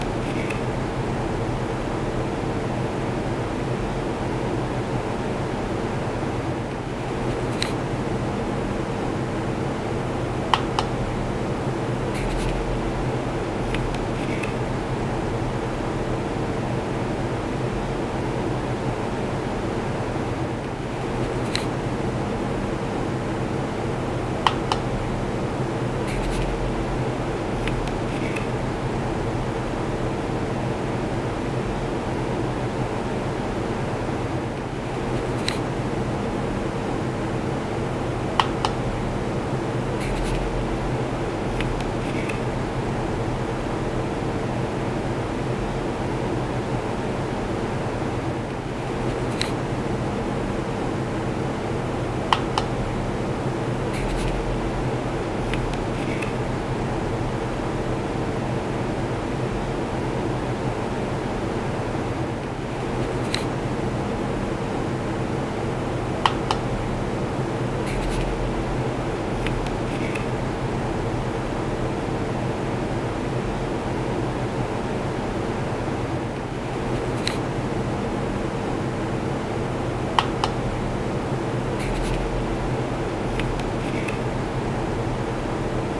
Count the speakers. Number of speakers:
zero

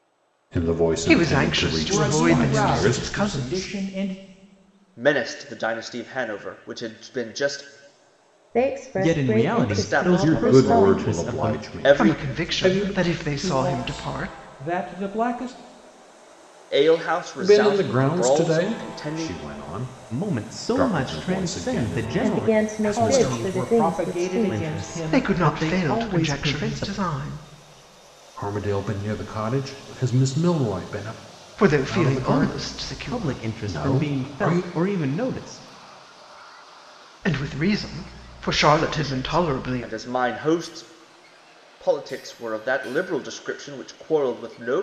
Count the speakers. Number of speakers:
six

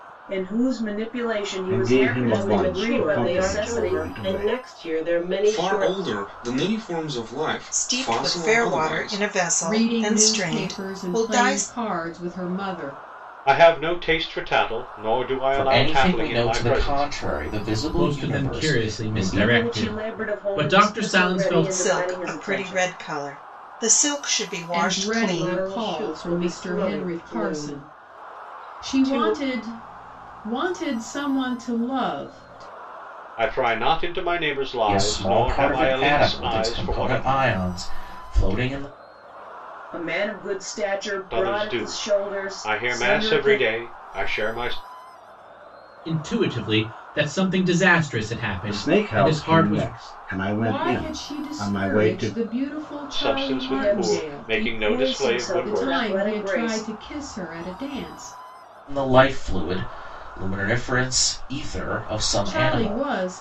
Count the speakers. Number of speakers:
nine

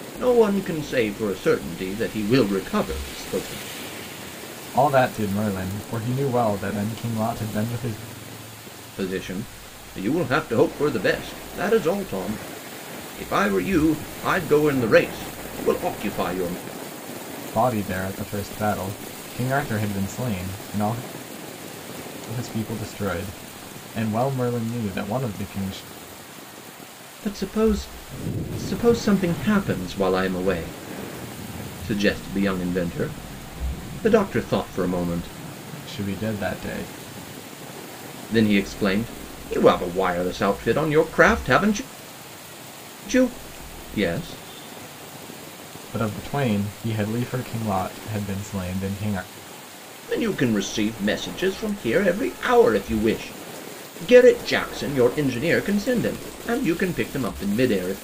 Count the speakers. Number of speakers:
two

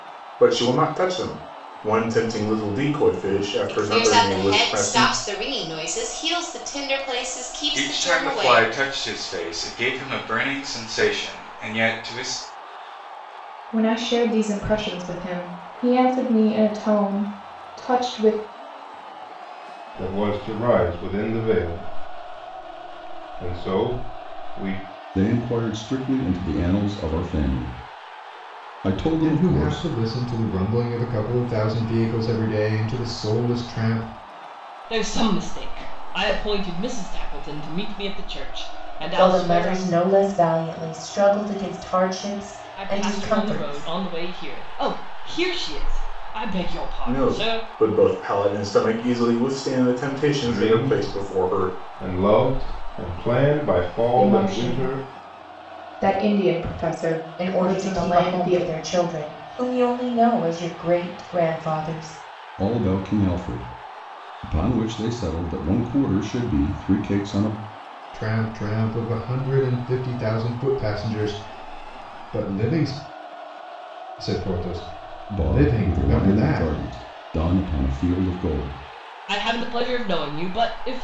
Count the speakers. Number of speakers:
nine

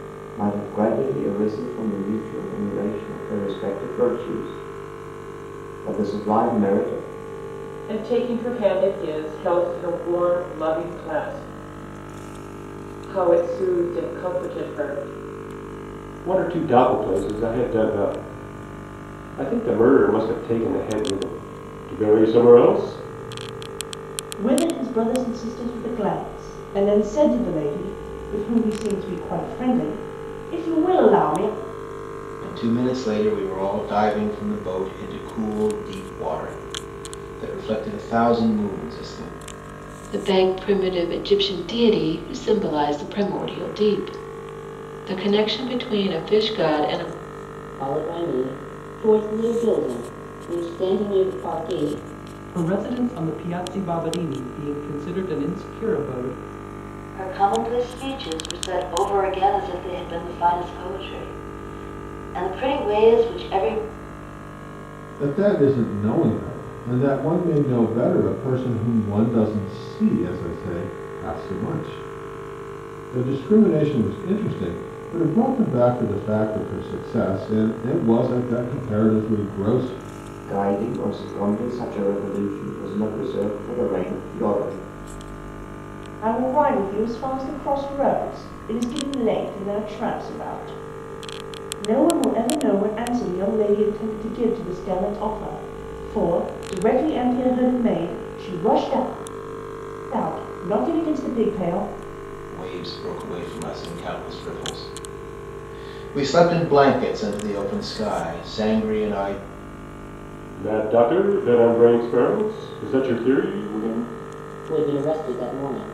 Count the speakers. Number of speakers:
ten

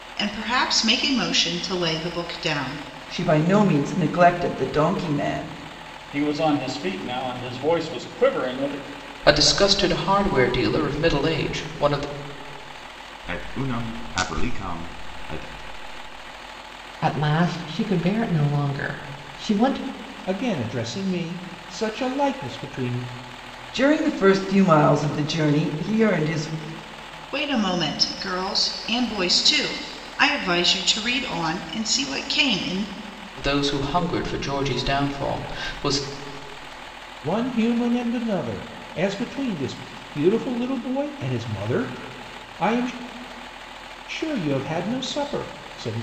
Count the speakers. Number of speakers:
seven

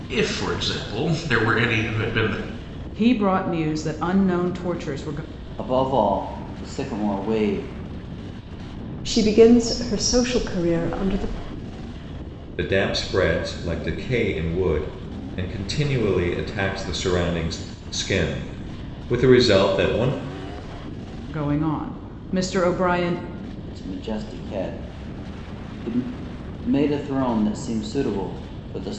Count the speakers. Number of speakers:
five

